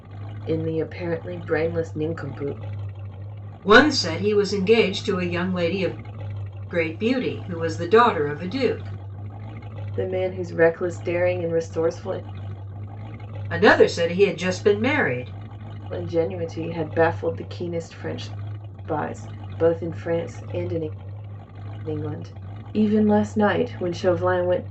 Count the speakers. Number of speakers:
2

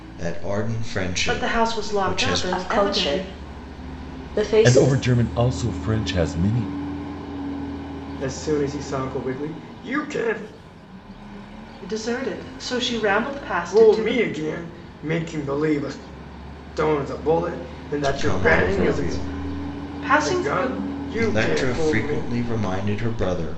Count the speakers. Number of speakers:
5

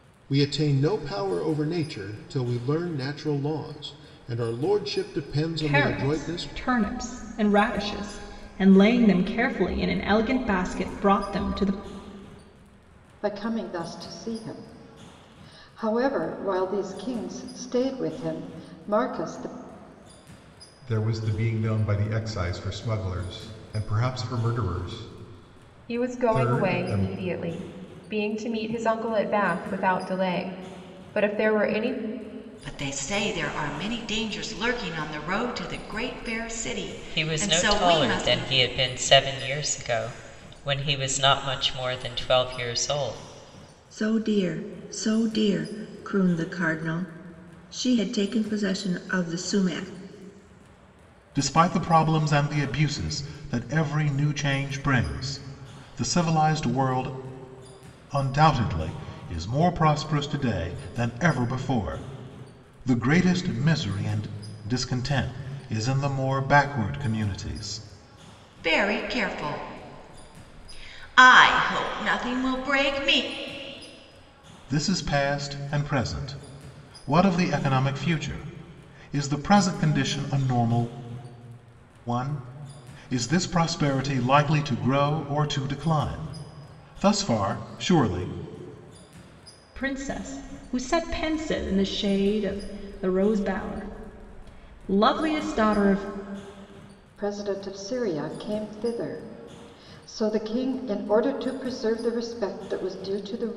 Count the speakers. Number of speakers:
9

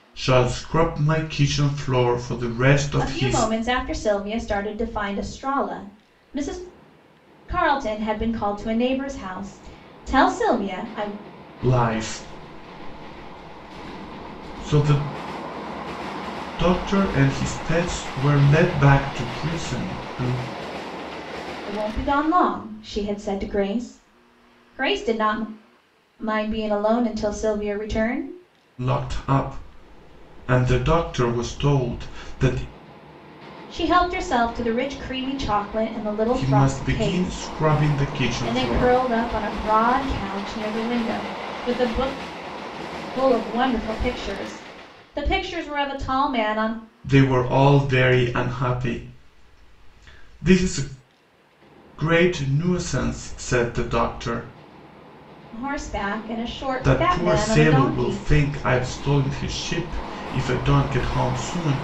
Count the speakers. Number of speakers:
2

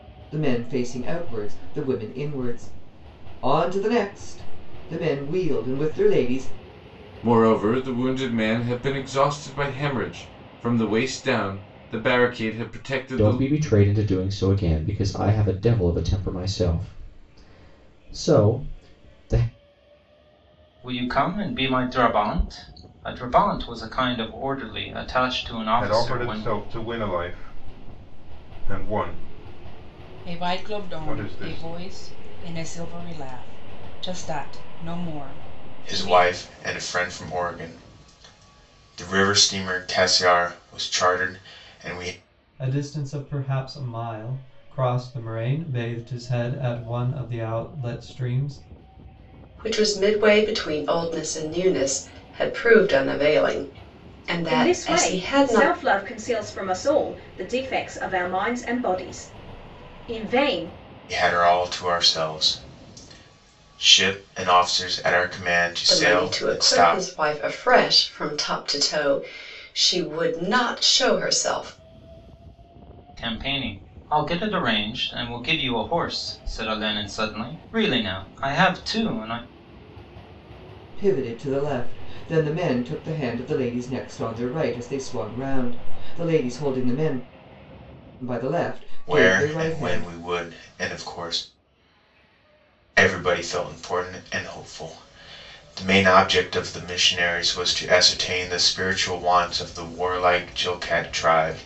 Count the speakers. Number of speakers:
10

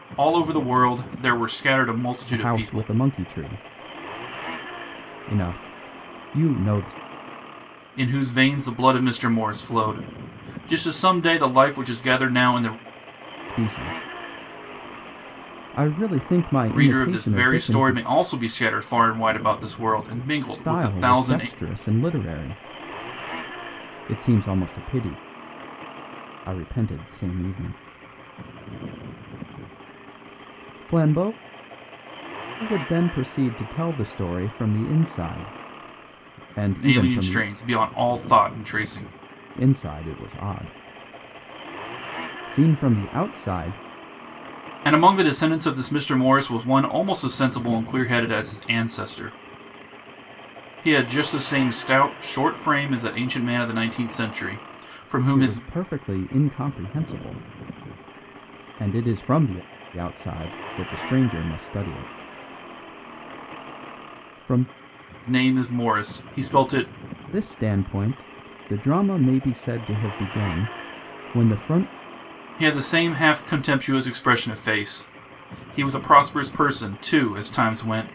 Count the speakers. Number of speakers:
2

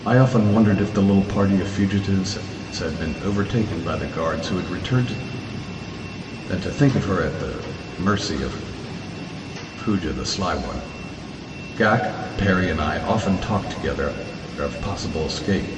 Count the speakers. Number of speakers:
1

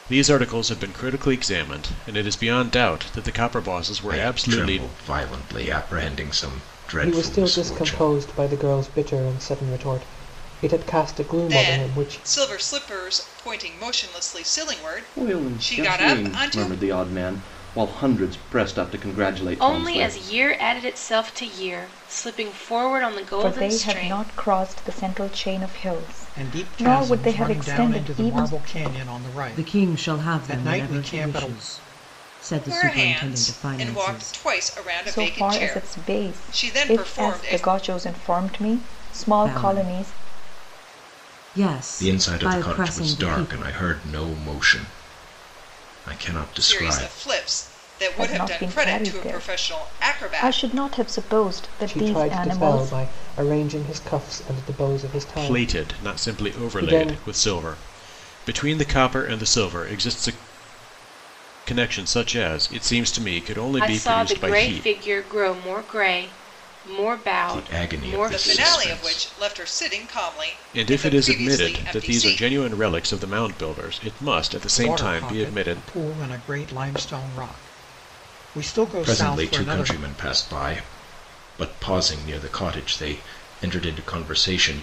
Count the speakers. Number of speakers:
9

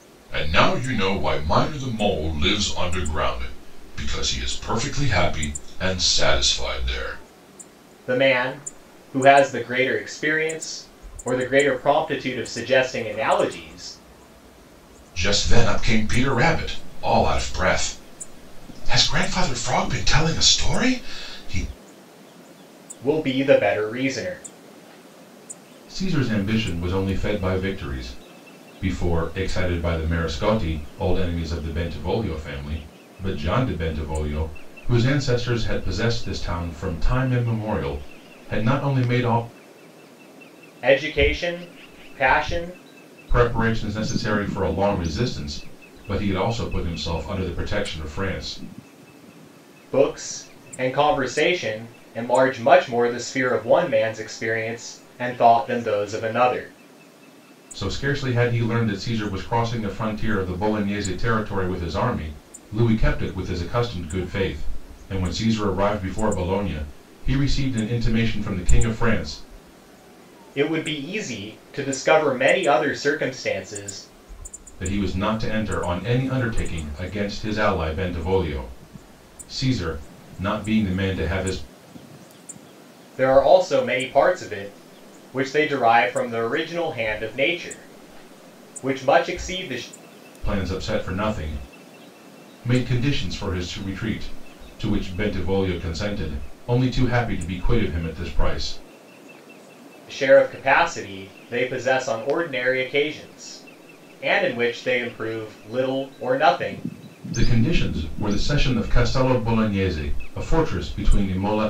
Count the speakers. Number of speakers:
2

